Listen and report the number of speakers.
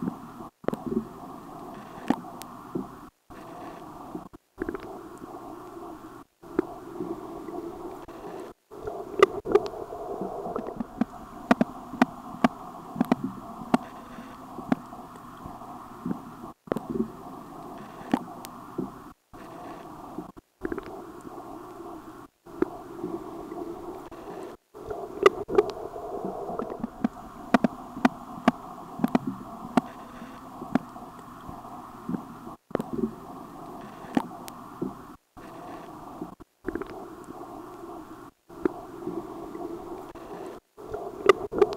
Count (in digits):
0